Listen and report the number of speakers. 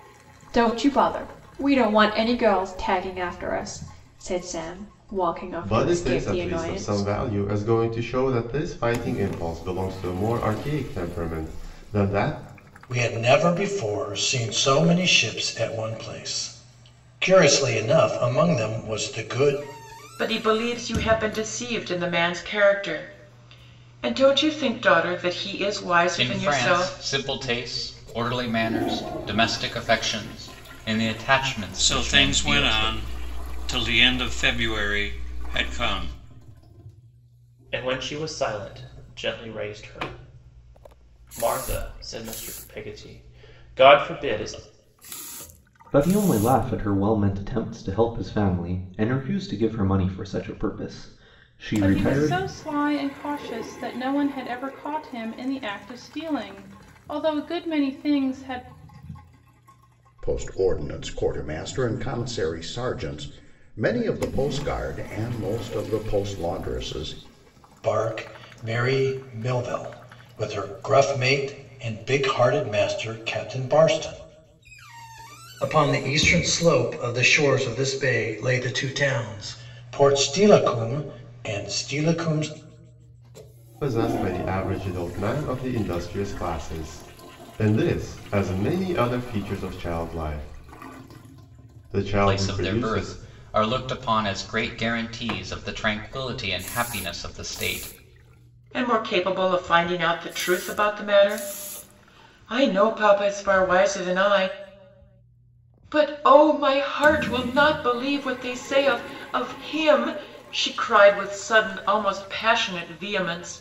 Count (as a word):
ten